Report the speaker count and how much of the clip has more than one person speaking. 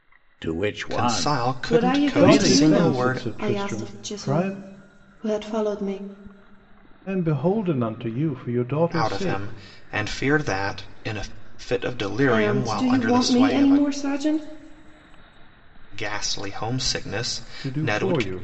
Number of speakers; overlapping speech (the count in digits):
4, about 36%